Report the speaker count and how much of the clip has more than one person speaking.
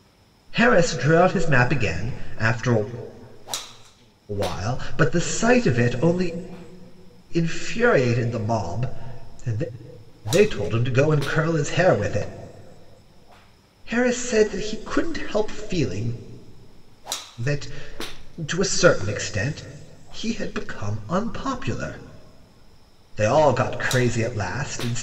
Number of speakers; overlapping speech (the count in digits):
1, no overlap